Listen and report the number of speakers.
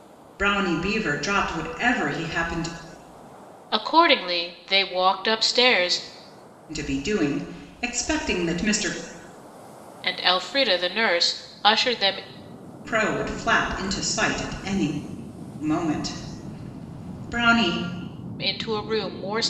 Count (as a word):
two